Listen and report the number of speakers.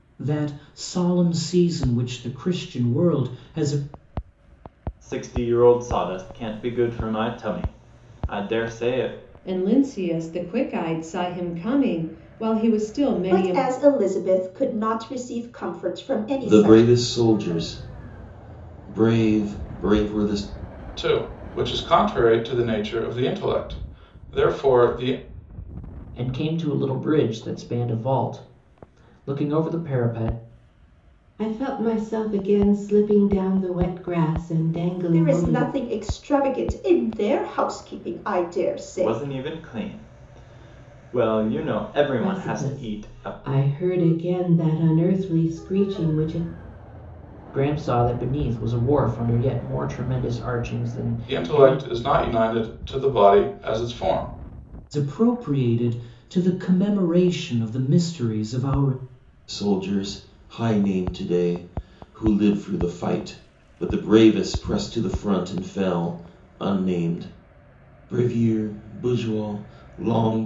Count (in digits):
8